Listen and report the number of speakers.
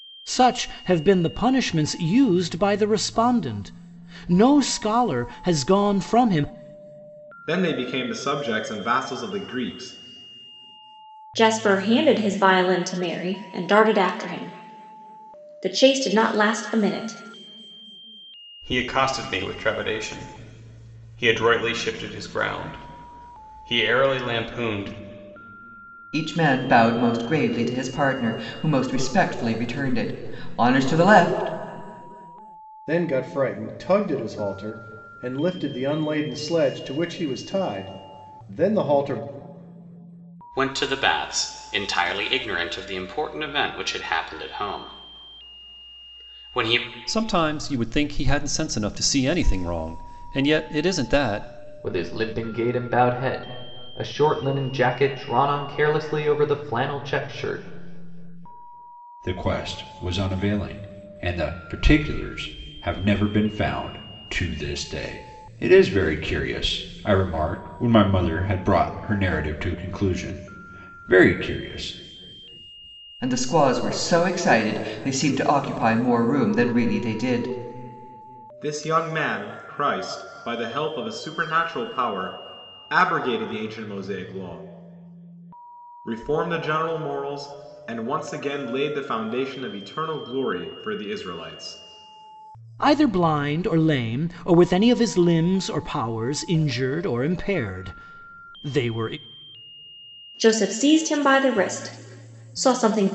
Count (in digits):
10